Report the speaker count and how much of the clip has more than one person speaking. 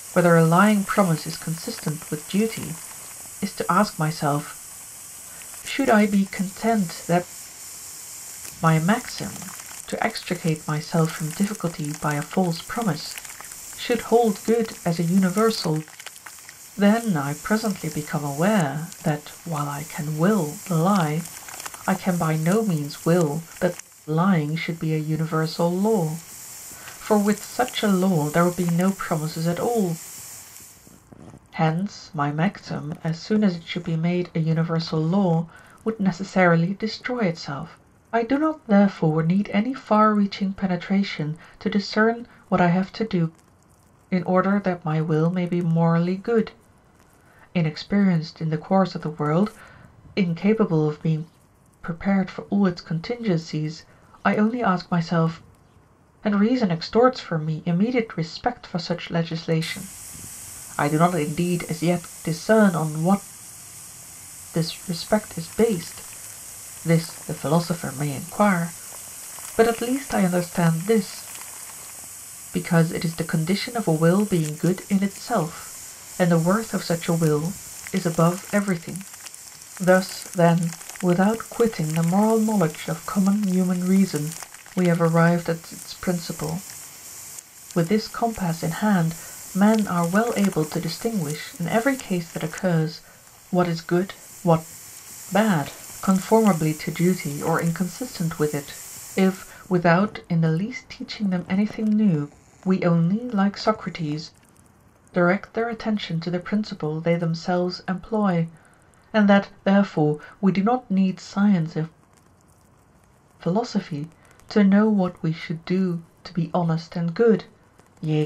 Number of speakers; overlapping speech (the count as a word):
one, no overlap